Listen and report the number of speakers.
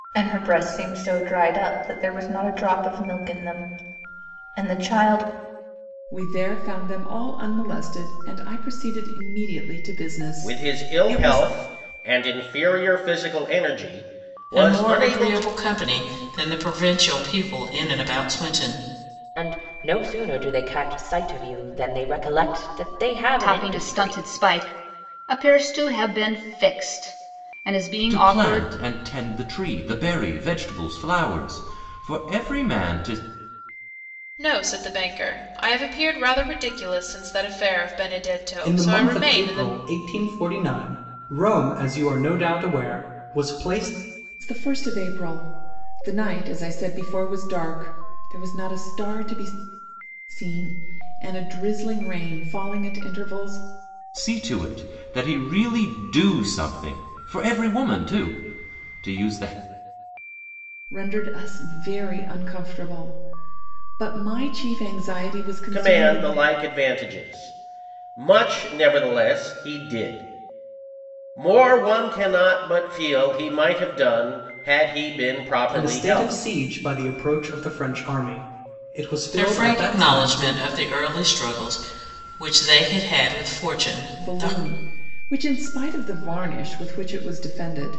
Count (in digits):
9